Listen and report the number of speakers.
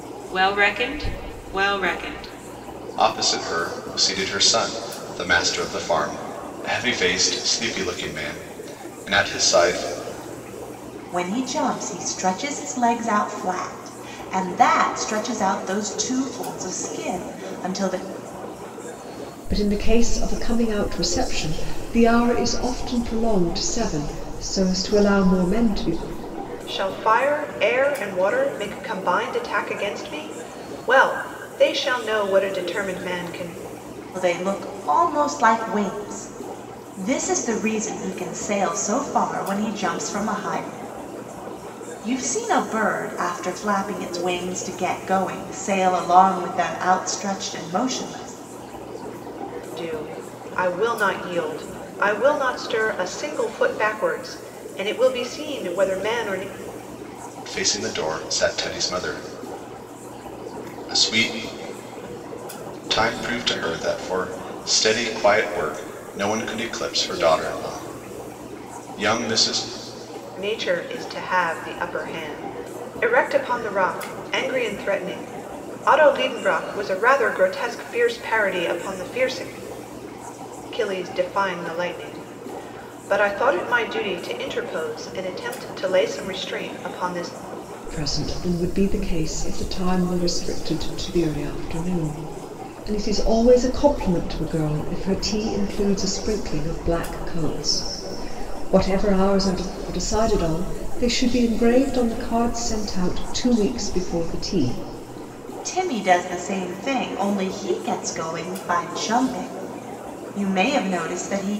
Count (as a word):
five